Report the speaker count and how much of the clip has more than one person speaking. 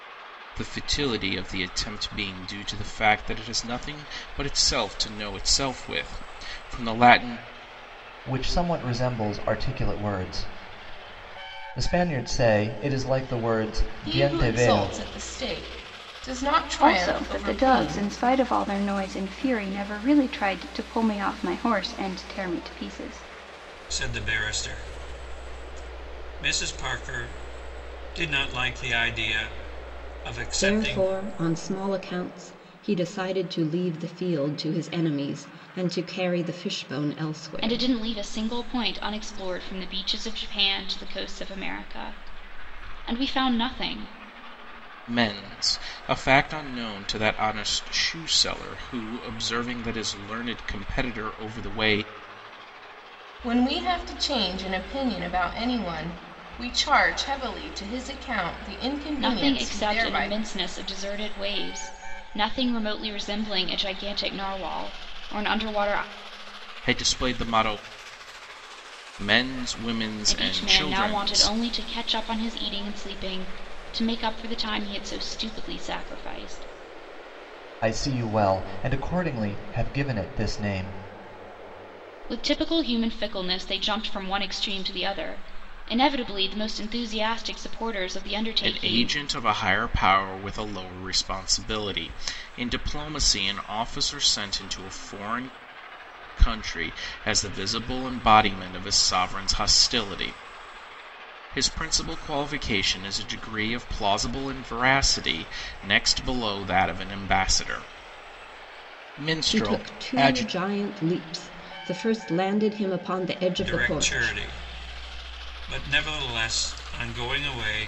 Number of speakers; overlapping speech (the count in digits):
7, about 7%